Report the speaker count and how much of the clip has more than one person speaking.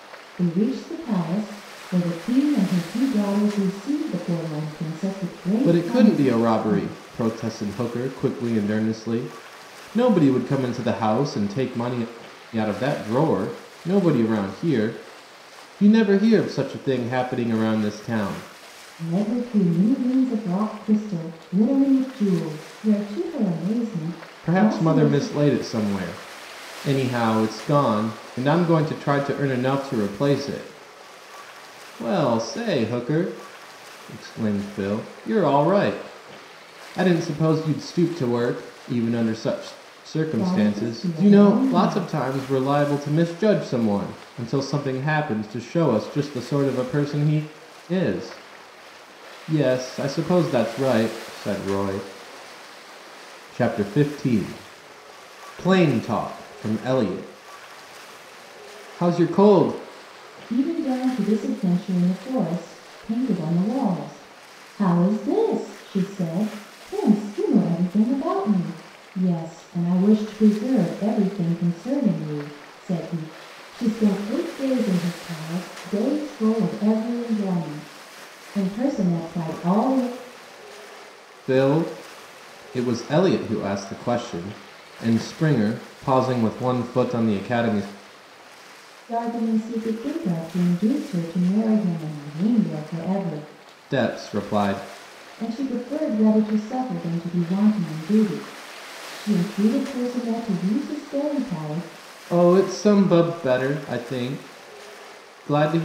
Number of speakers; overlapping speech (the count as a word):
two, about 4%